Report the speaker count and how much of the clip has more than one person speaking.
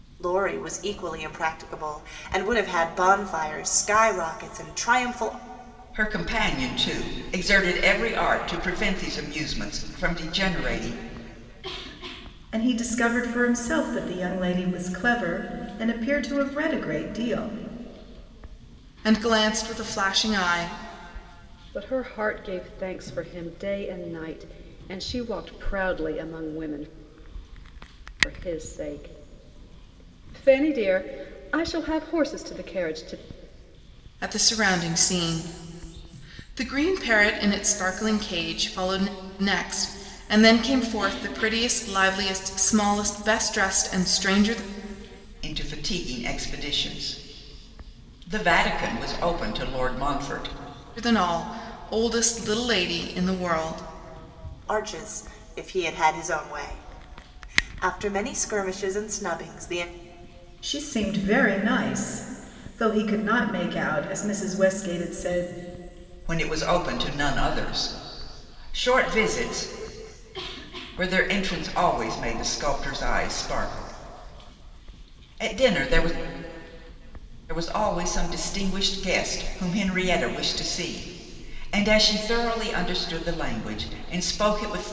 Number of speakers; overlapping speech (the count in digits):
5, no overlap